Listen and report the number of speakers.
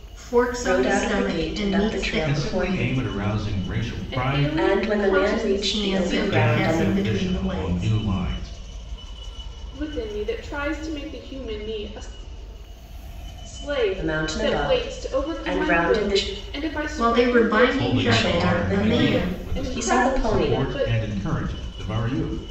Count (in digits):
4